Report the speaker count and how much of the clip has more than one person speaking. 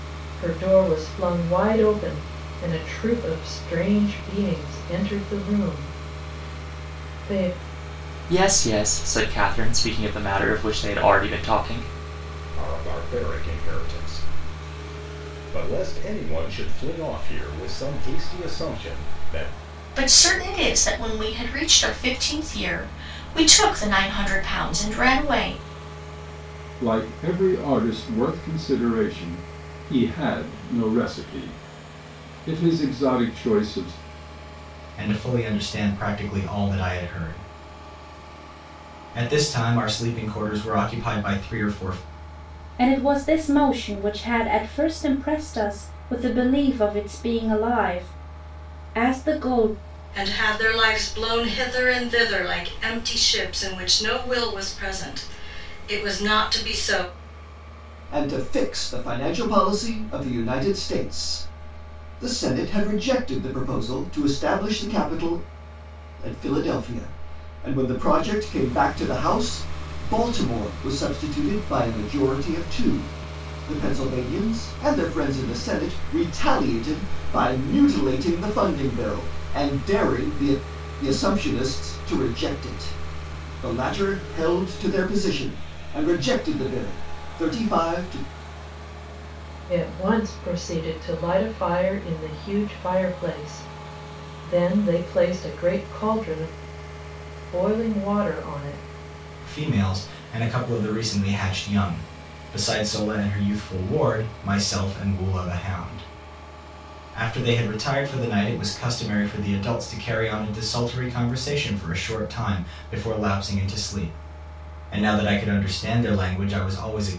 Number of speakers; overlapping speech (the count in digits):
9, no overlap